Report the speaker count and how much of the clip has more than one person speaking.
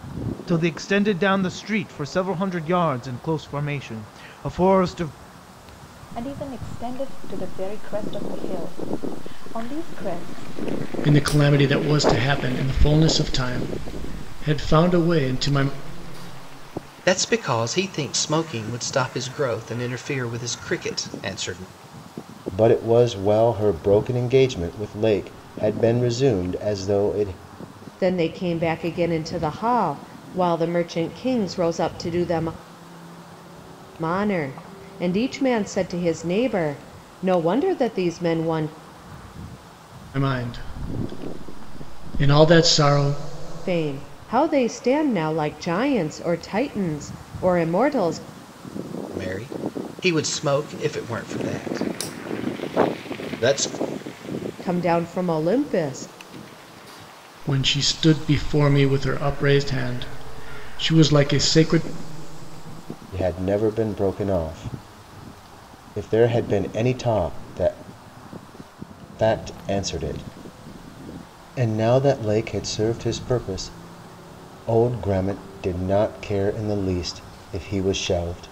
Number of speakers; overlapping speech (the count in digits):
6, no overlap